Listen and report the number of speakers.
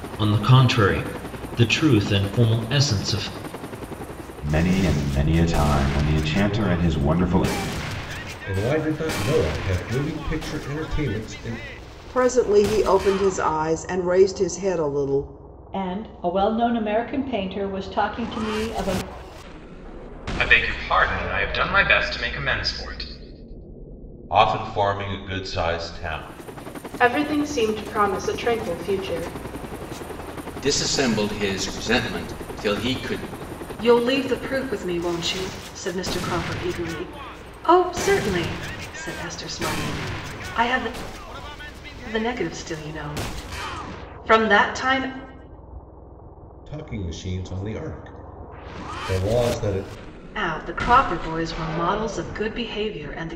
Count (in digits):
10